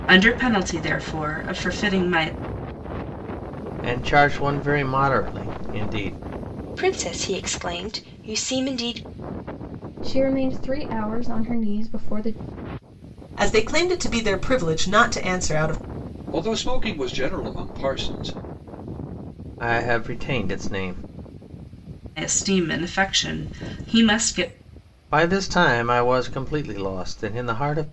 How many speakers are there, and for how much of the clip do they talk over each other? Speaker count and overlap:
6, no overlap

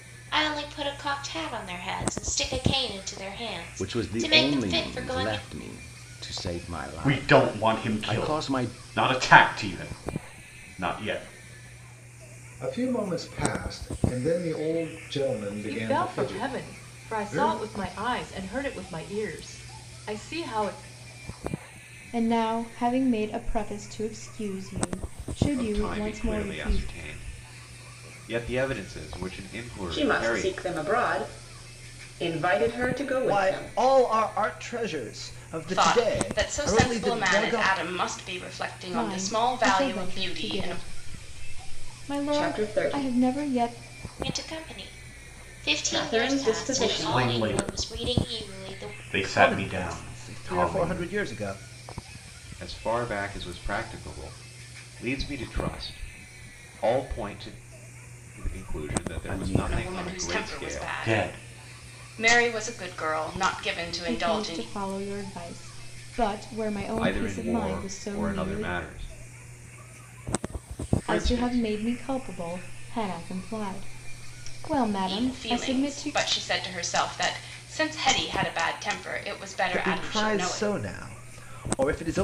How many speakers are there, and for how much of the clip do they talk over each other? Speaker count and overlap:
10, about 34%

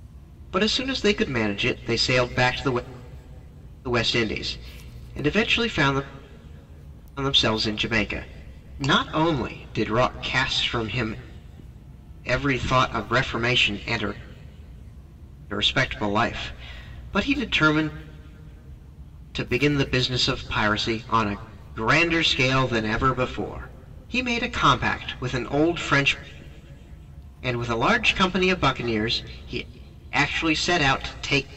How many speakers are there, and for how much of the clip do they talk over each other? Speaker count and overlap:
1, no overlap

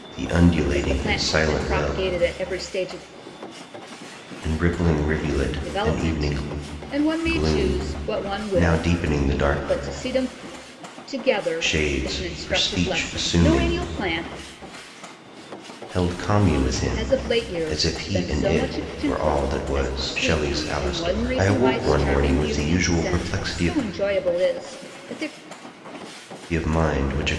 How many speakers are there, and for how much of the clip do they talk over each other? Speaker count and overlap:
2, about 50%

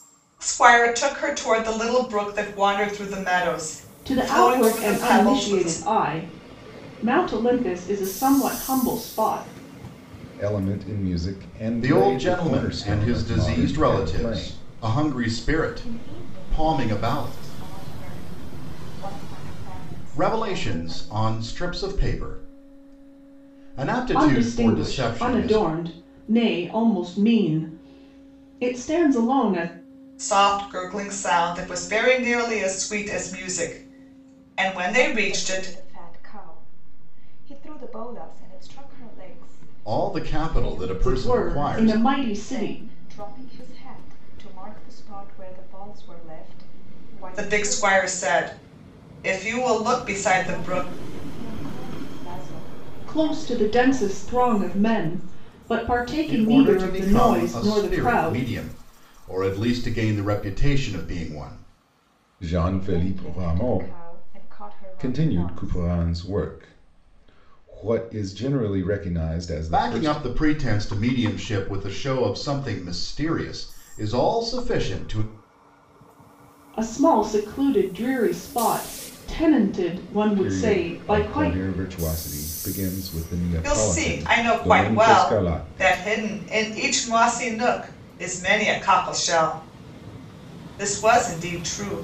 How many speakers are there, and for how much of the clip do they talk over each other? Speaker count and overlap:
5, about 27%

